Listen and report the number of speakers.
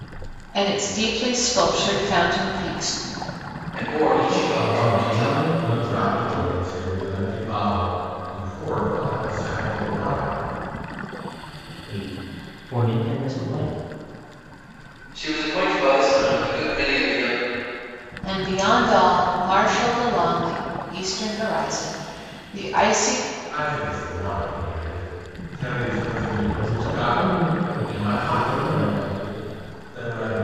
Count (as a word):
four